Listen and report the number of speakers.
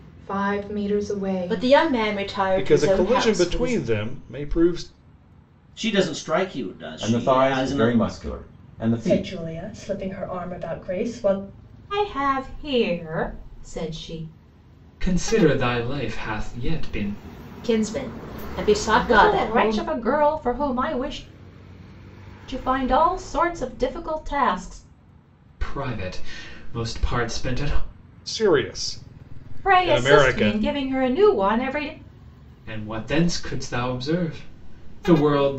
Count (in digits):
8